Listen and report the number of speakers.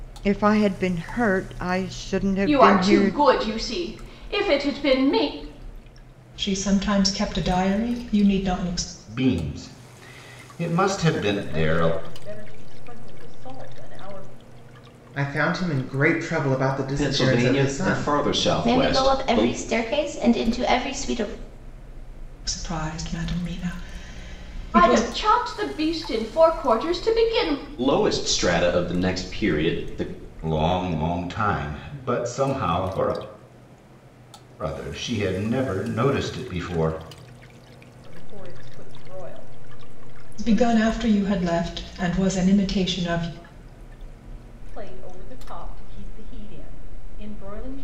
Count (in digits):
8